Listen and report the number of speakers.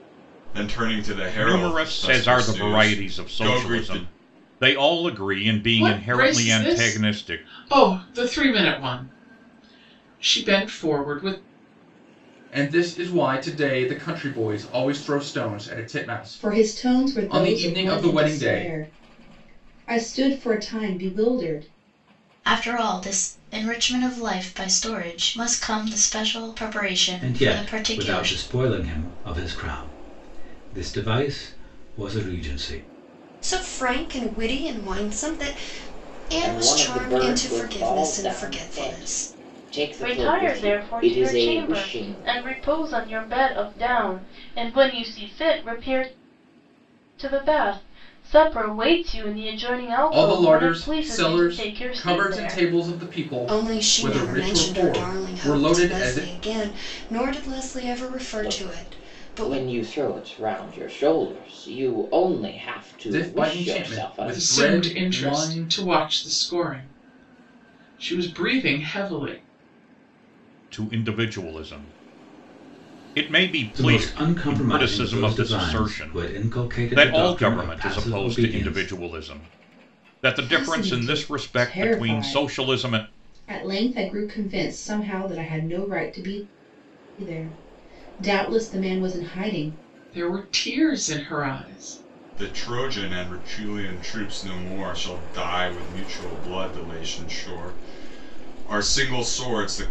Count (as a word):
ten